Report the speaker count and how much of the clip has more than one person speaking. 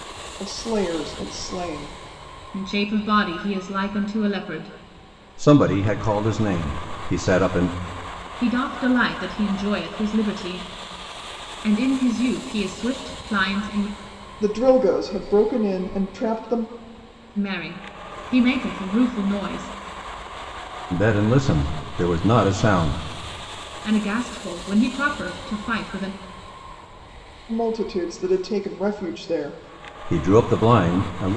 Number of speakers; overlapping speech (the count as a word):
three, no overlap